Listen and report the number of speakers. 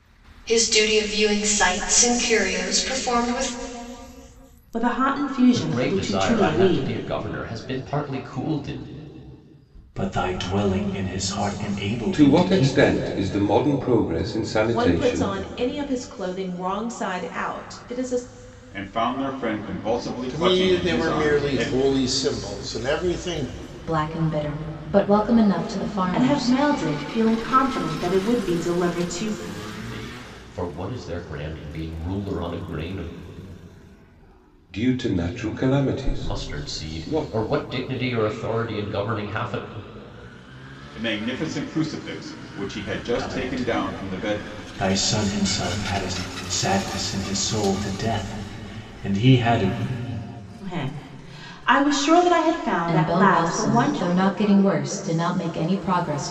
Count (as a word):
nine